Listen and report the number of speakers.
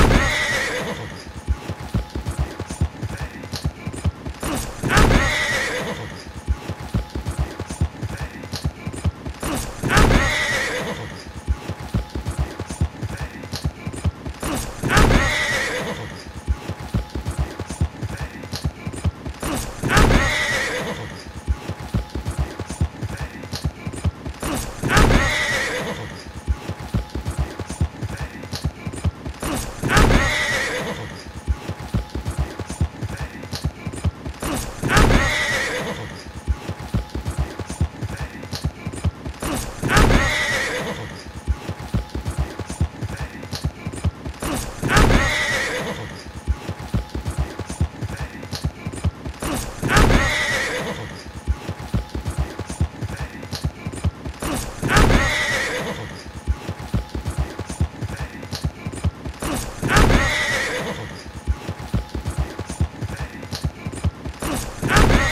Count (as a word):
zero